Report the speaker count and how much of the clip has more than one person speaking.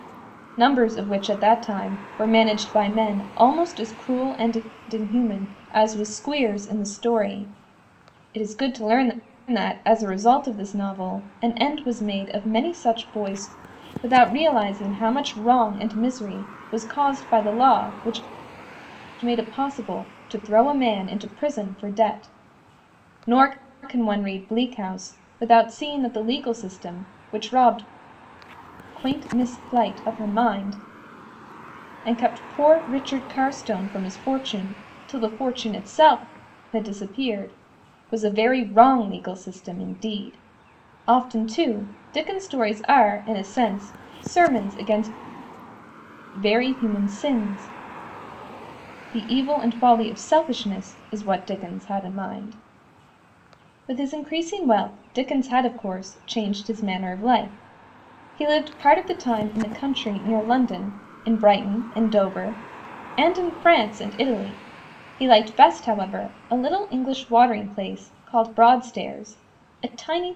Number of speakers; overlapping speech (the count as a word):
one, no overlap